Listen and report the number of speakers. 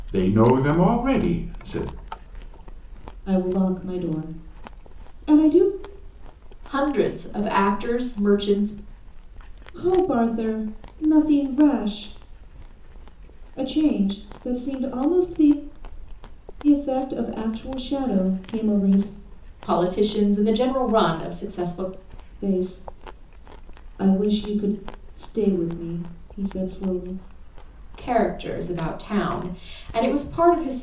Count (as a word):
three